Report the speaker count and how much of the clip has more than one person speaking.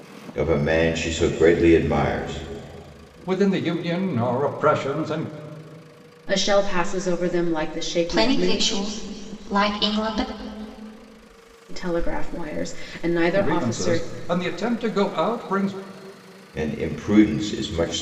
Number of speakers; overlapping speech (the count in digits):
4, about 8%